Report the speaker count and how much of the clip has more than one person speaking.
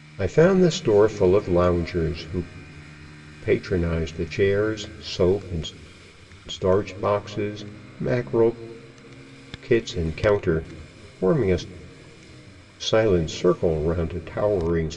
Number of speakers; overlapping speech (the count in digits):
1, no overlap